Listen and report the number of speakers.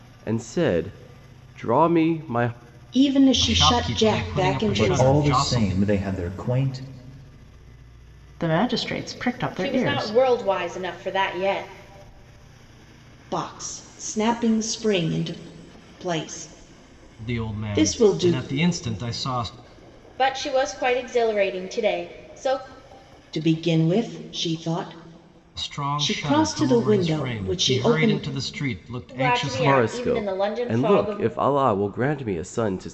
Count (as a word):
six